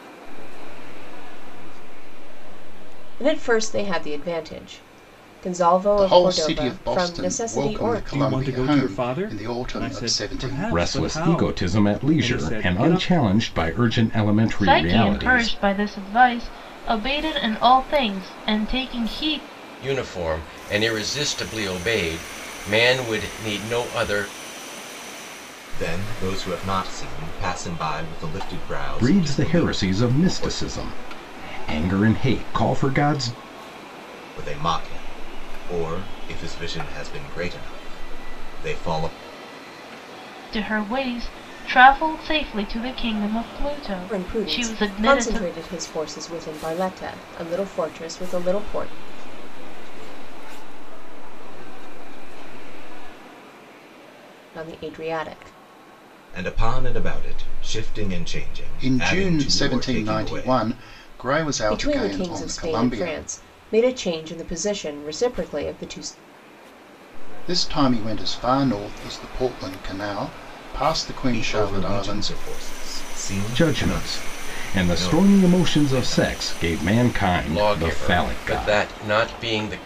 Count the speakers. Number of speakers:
8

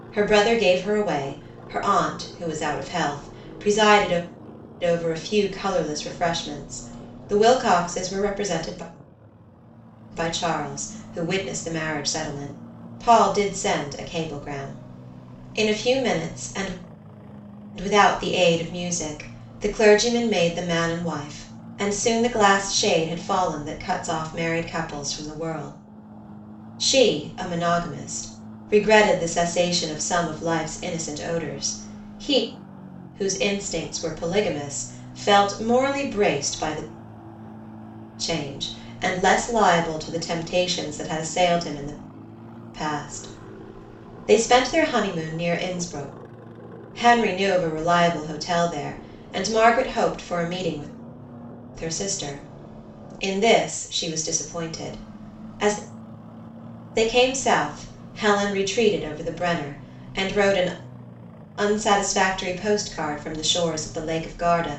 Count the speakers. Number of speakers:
1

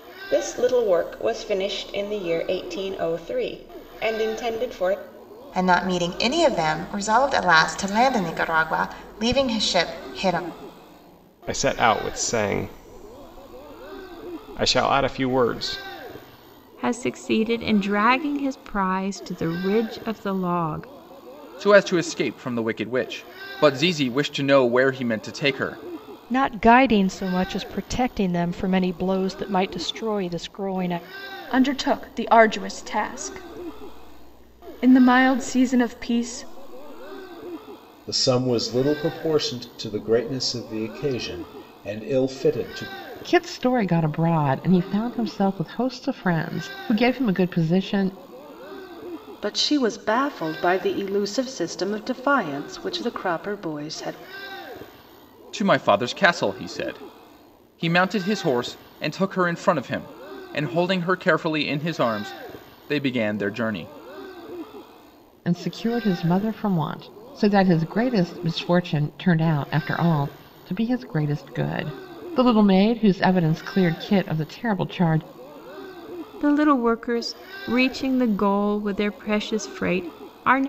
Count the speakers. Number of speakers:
10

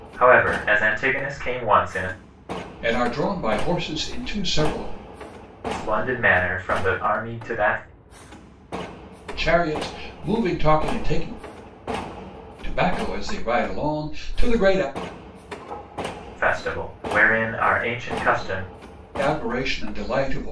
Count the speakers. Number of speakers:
2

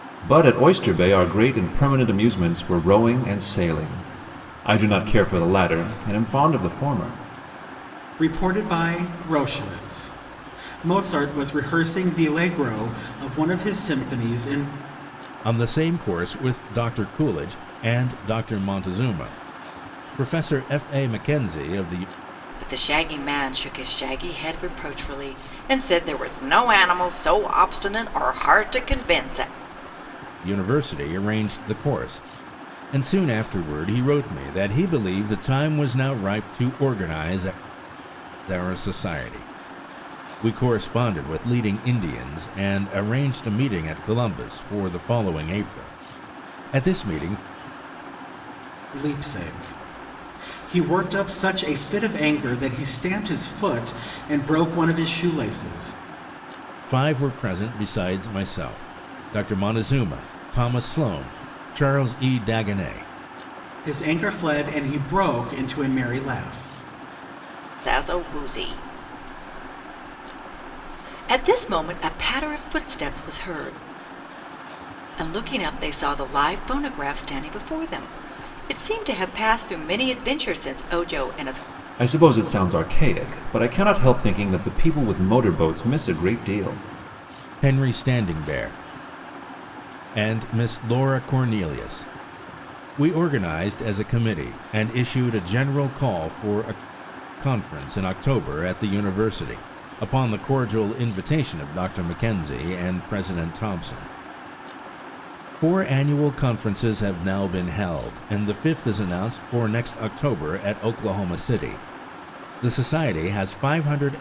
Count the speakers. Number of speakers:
4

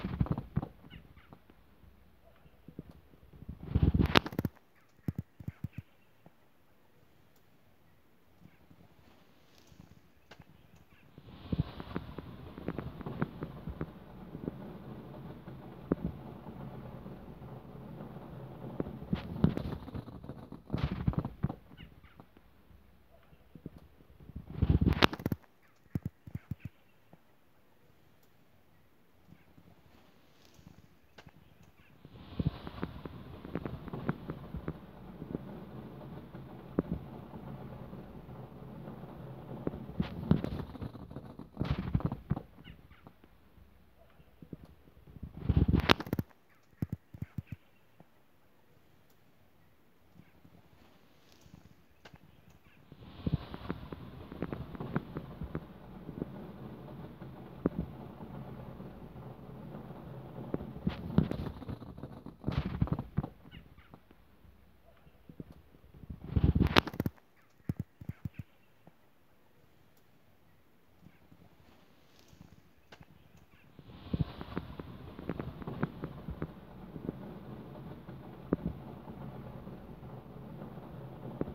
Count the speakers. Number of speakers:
0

